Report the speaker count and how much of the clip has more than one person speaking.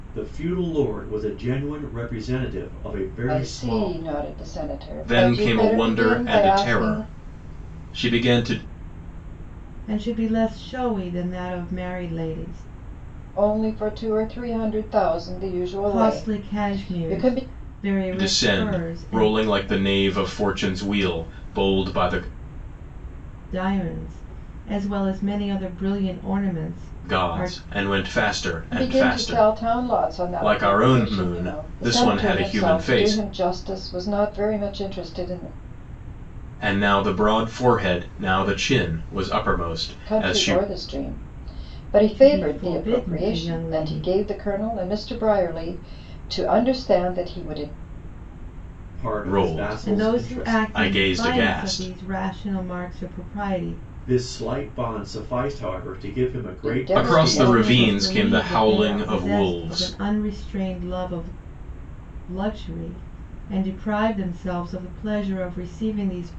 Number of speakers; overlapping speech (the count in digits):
4, about 29%